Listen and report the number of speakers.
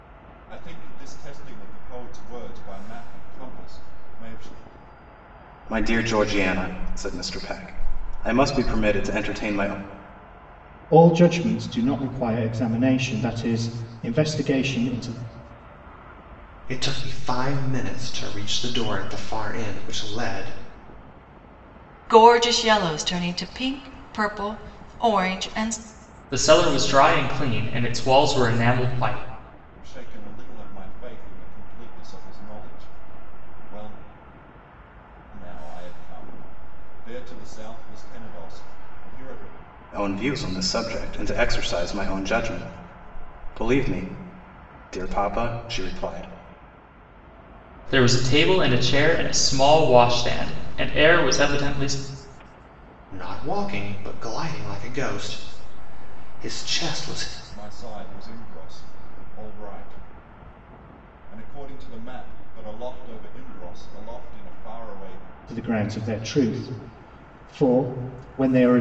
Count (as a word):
six